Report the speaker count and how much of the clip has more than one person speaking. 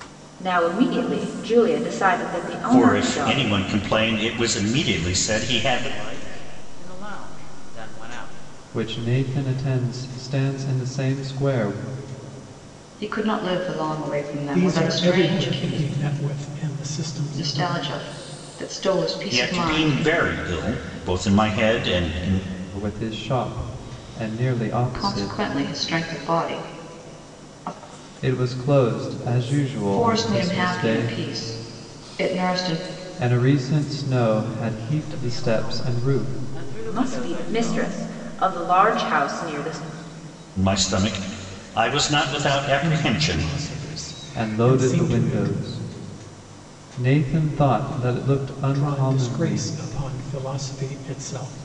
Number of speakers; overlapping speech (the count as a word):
six, about 23%